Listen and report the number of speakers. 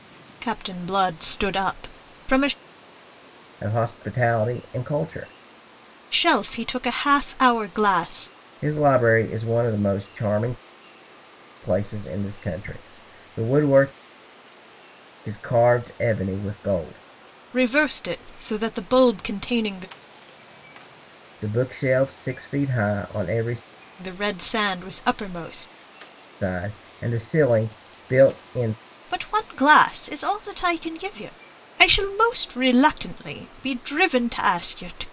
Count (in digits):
2